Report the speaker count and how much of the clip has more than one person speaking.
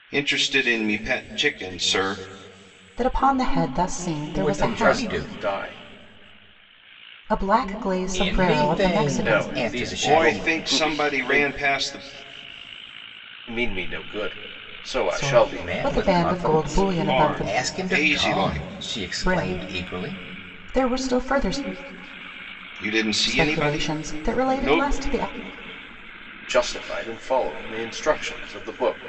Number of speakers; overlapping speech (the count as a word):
four, about 36%